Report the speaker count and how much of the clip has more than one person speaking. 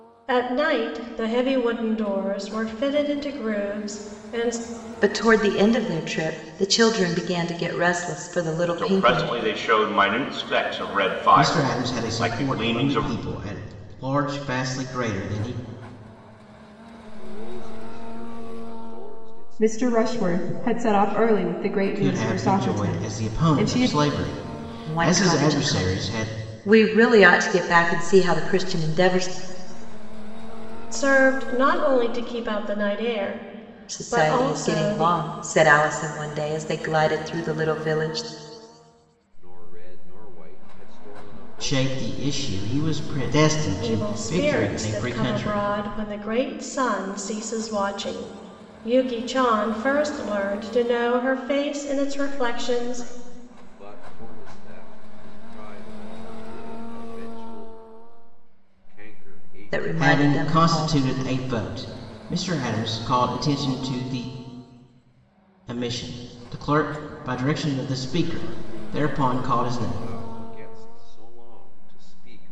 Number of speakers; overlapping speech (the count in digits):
6, about 29%